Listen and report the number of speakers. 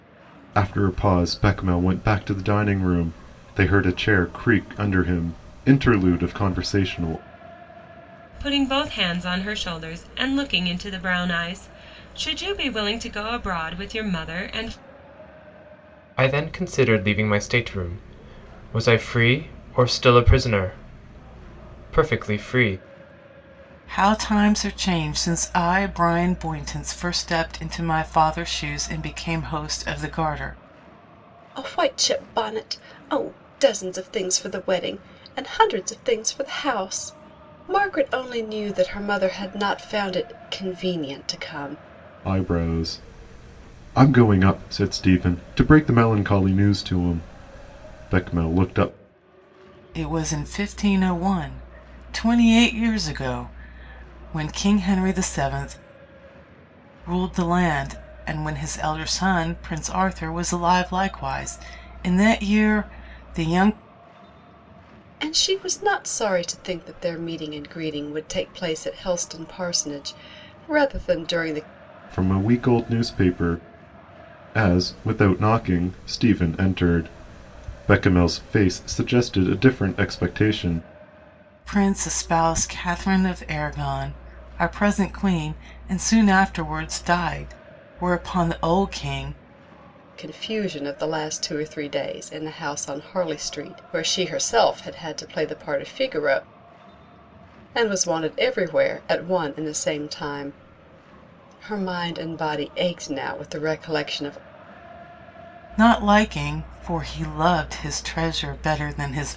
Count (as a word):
five